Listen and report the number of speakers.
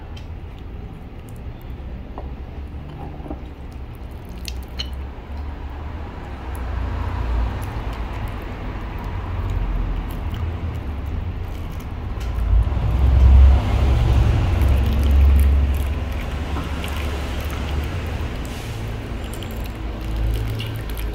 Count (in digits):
0